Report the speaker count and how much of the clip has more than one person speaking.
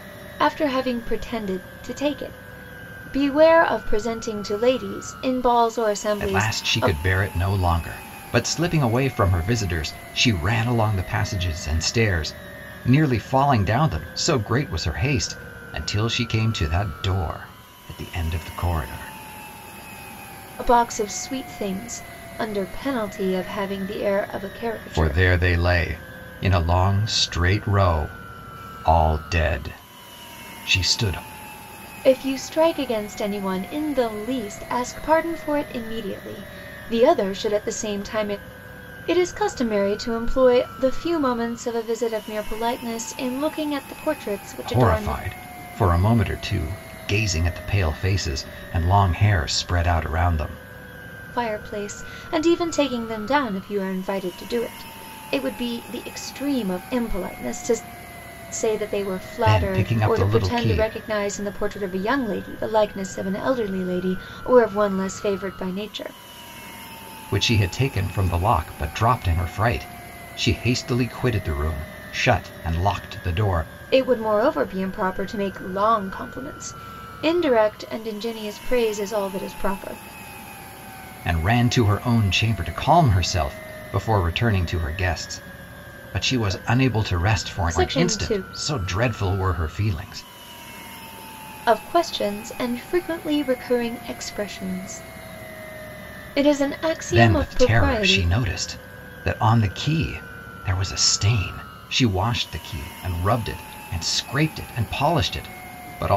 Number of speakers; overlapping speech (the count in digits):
2, about 6%